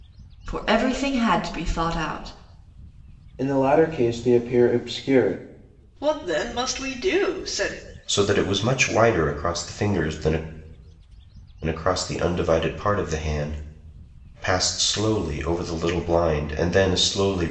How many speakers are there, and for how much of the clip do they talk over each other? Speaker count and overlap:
4, no overlap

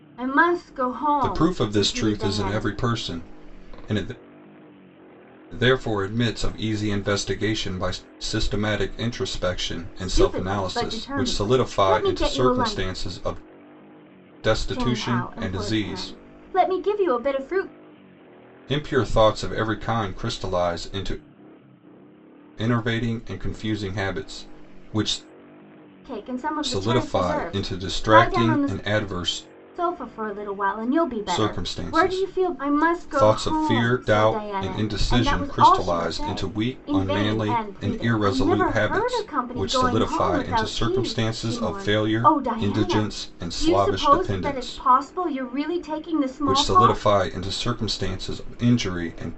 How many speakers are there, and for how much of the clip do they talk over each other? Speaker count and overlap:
2, about 44%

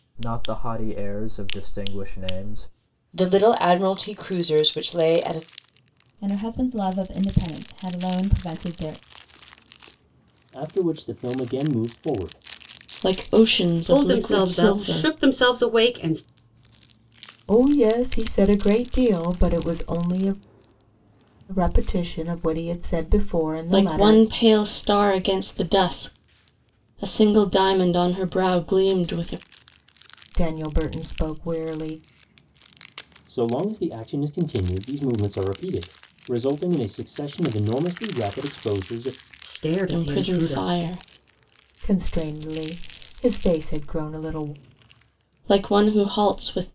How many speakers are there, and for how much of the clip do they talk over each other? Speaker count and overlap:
7, about 6%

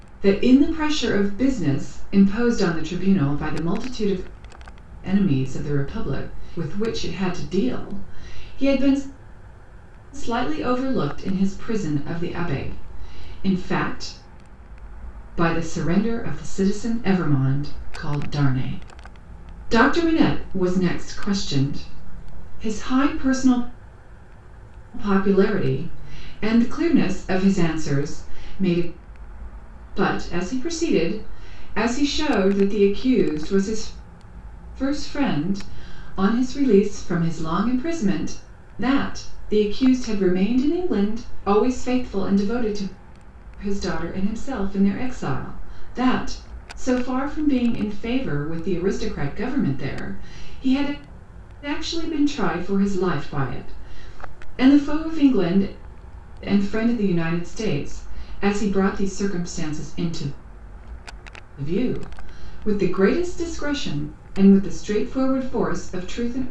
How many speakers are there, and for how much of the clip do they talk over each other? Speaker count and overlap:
1, no overlap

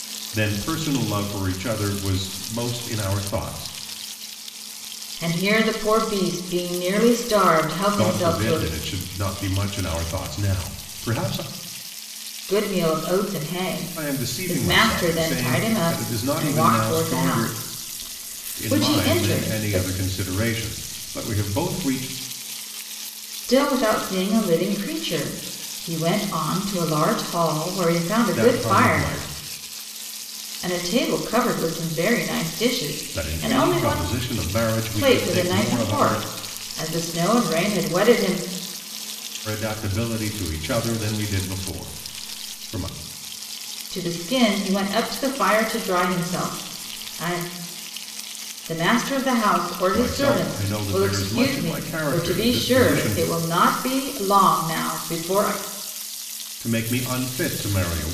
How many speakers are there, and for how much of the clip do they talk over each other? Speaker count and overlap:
2, about 20%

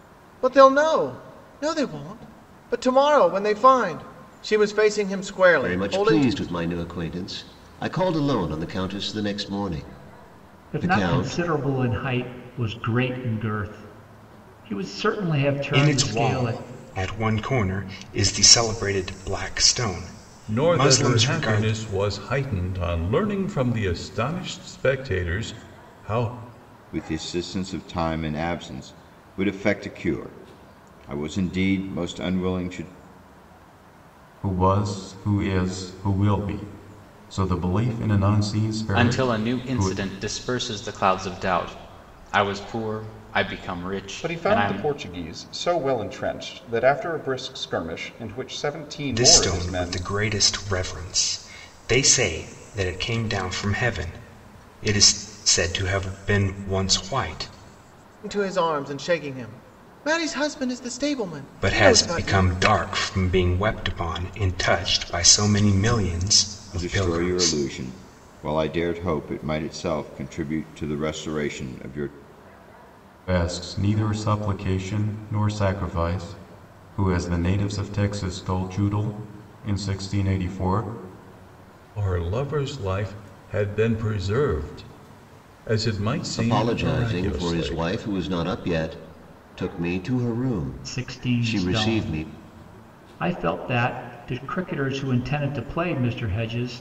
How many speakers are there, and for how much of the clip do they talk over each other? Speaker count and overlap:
9, about 11%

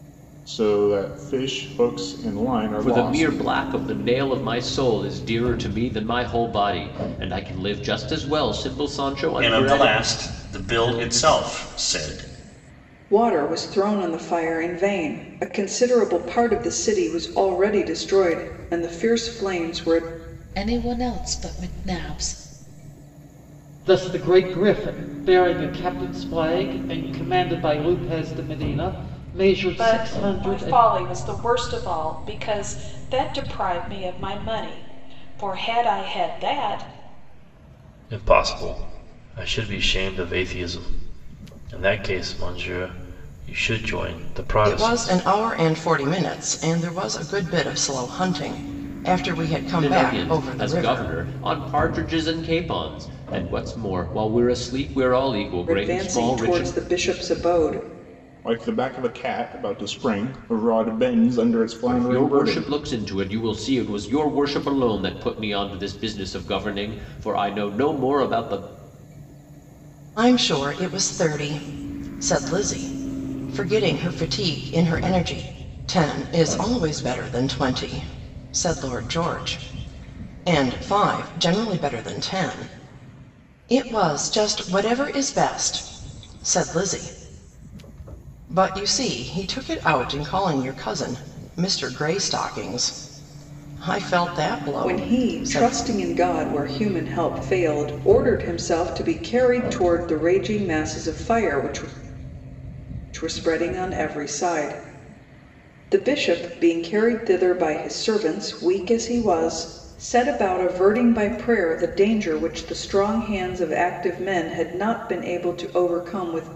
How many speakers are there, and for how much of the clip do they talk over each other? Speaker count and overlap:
9, about 6%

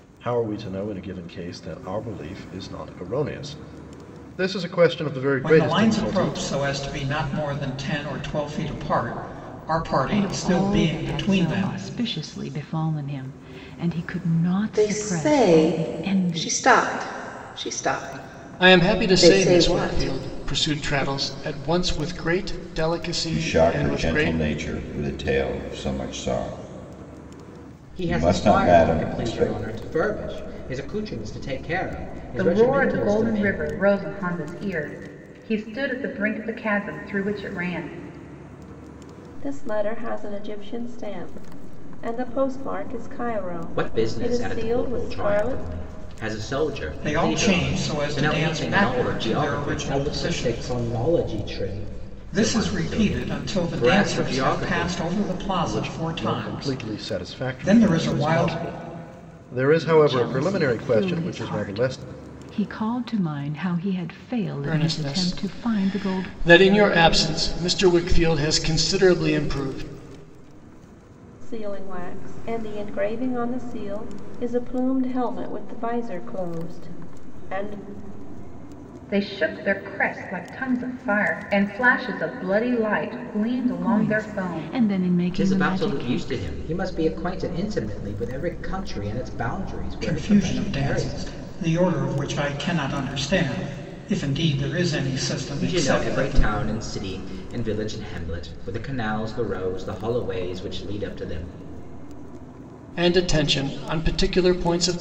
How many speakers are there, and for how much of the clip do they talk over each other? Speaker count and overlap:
9, about 30%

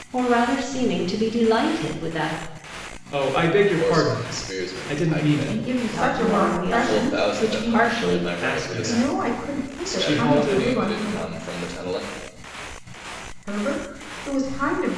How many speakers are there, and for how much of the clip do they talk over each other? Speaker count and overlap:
4, about 50%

